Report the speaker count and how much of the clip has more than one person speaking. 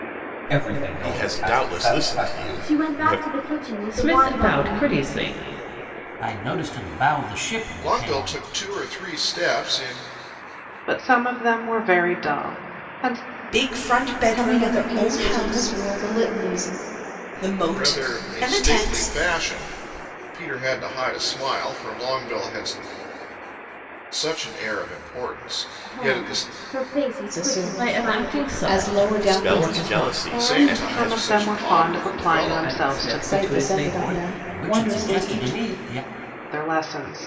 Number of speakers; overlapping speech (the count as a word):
nine, about 43%